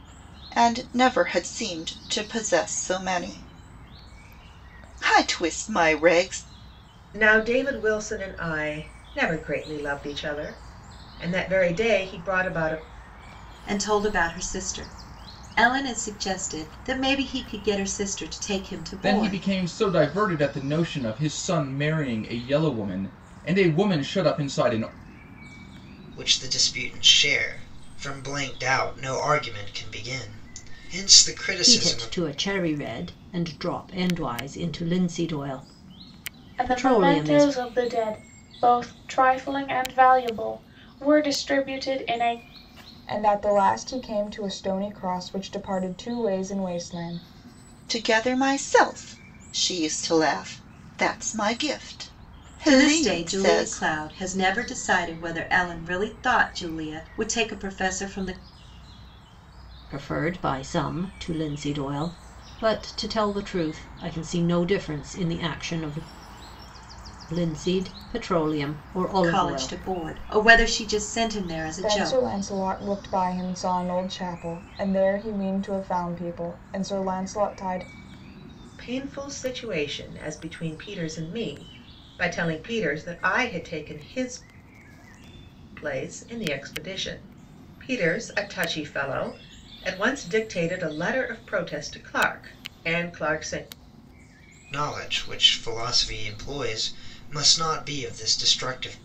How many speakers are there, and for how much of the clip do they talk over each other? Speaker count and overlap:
8, about 5%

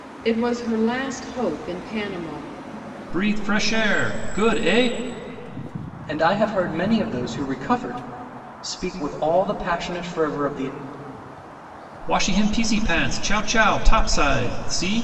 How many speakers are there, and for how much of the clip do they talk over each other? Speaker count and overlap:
3, no overlap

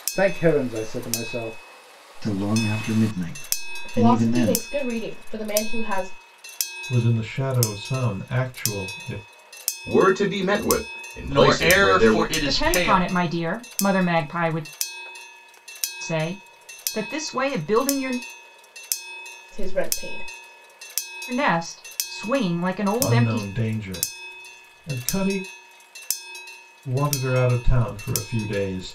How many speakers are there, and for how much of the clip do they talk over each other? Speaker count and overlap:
7, about 10%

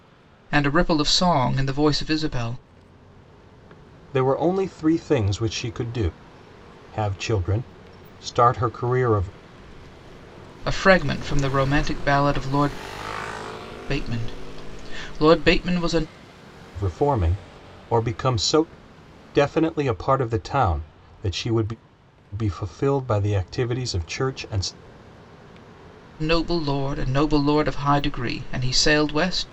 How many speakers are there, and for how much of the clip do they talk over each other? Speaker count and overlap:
2, no overlap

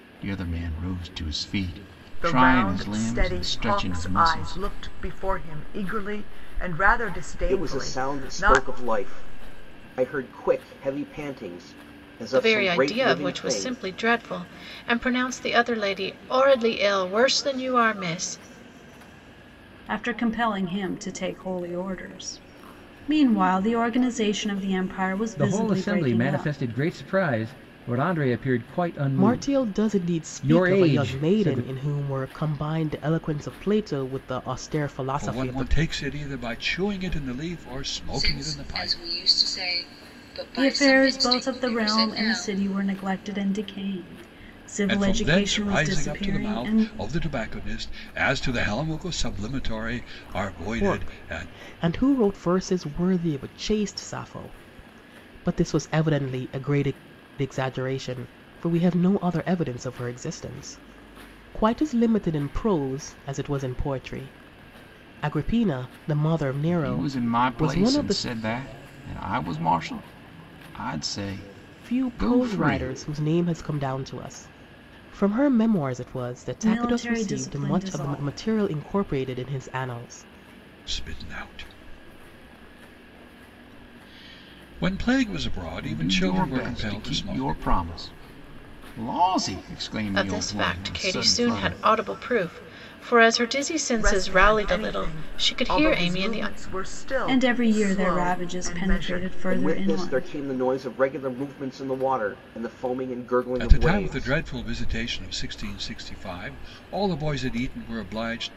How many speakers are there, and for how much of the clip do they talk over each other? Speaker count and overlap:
9, about 29%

